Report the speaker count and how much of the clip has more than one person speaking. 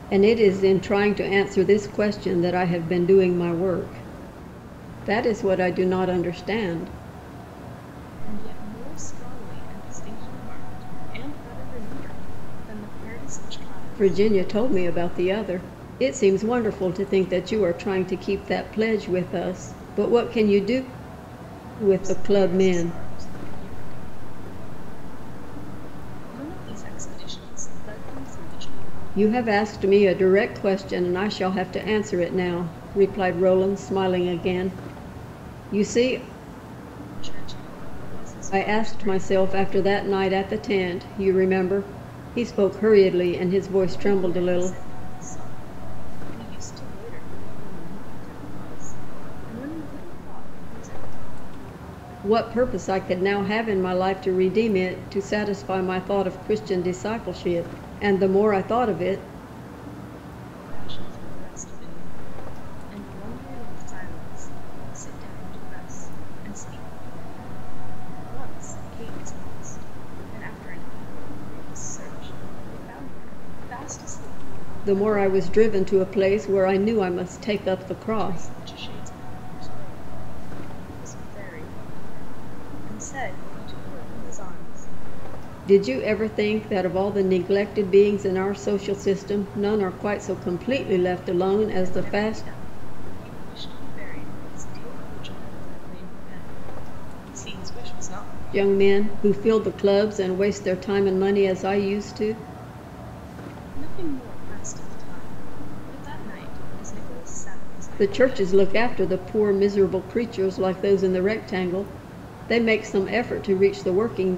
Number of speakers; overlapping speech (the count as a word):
two, about 6%